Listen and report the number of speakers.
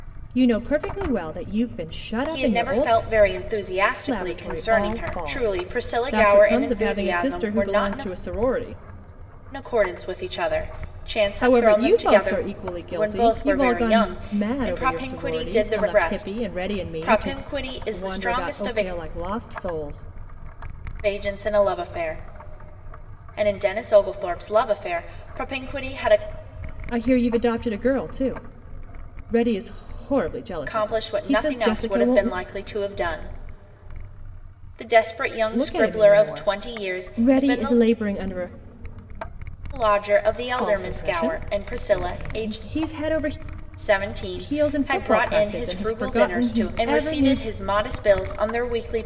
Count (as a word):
two